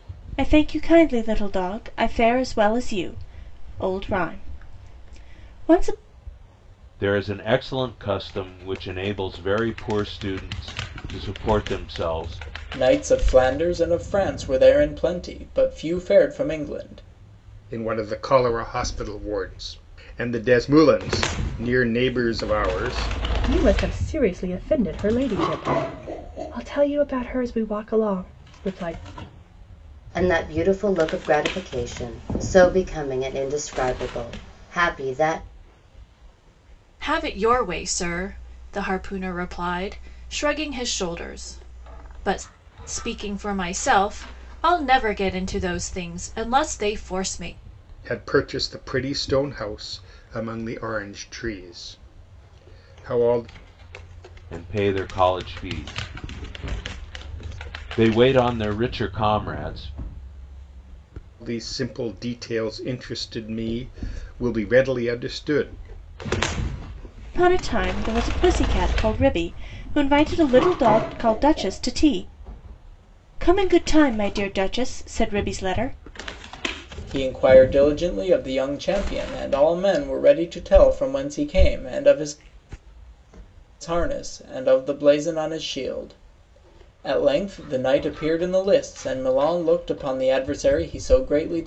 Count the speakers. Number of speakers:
seven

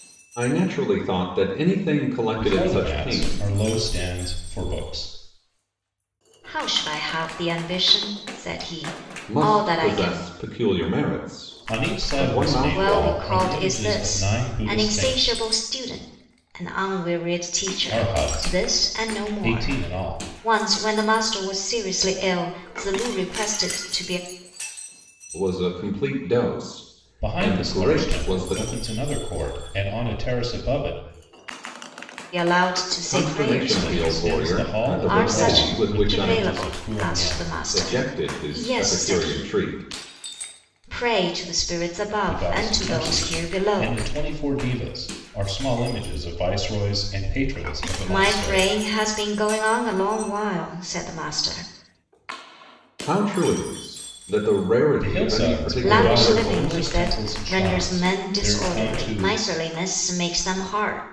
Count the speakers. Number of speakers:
three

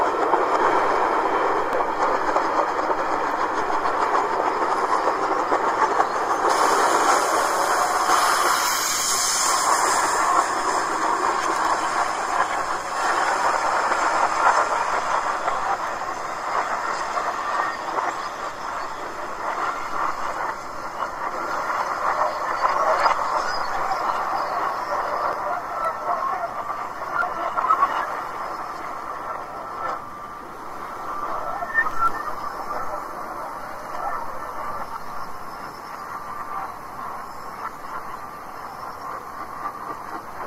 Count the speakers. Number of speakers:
zero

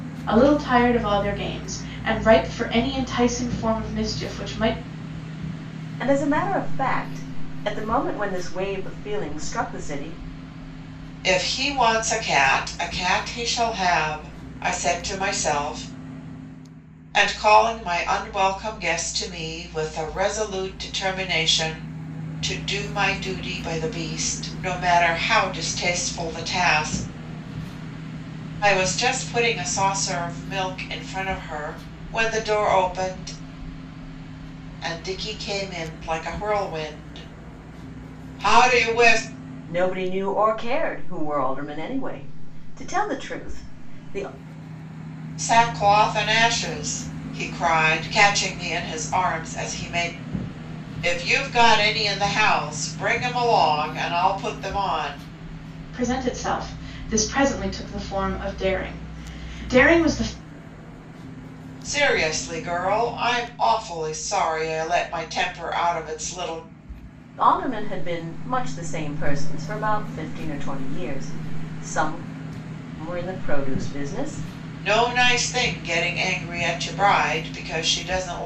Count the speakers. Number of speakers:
three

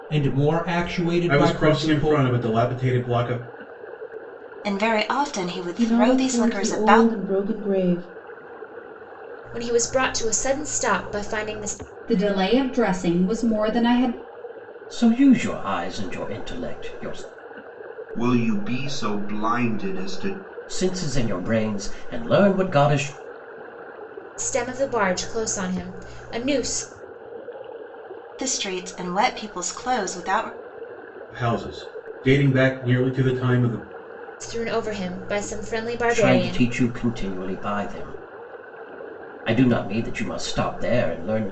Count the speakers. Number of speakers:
eight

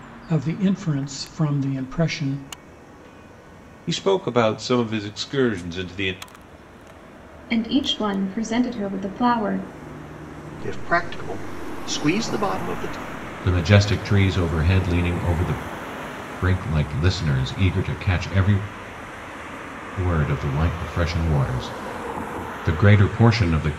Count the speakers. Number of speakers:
five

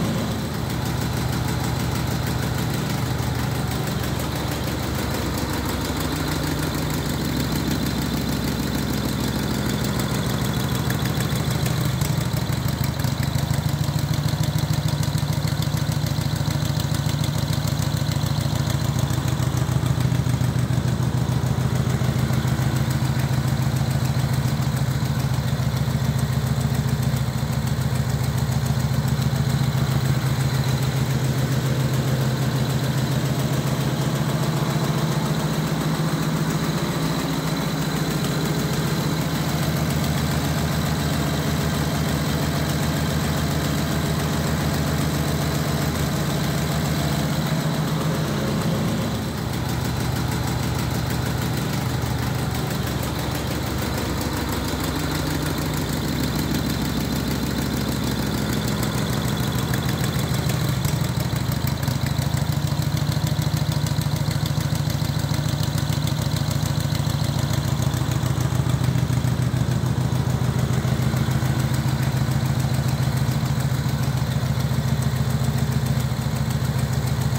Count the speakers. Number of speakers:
zero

